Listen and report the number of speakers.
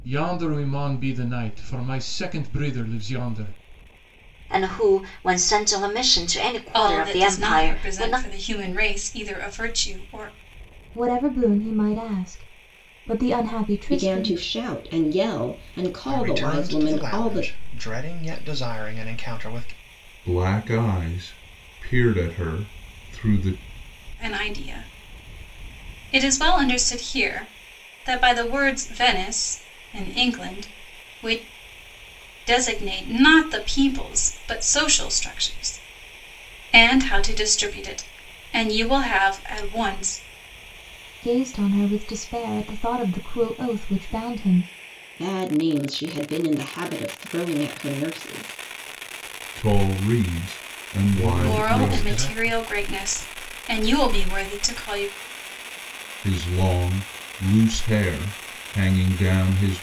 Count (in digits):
7